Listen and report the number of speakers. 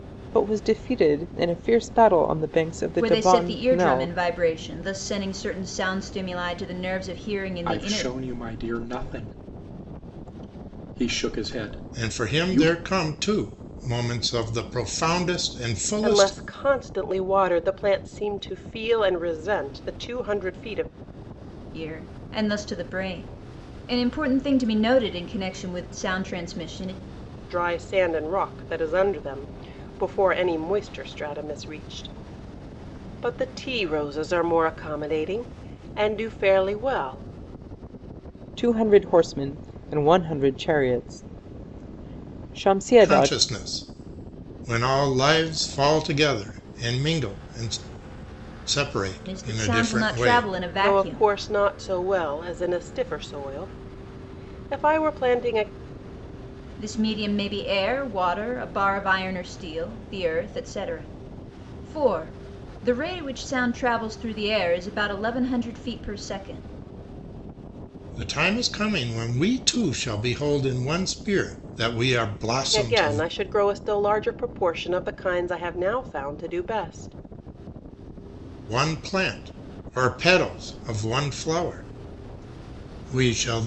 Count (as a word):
five